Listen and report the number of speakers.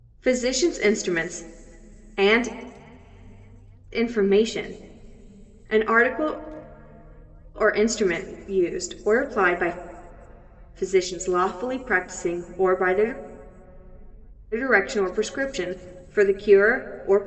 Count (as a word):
one